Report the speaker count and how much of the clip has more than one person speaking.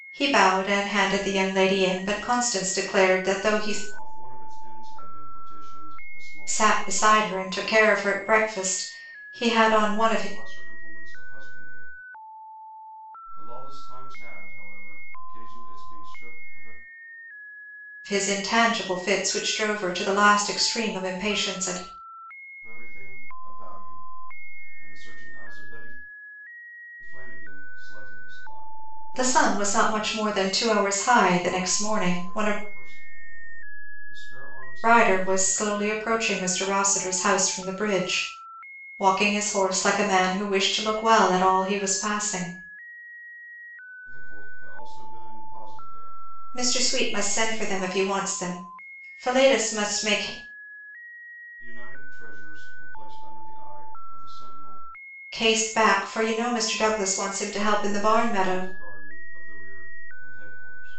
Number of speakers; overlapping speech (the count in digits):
2, about 11%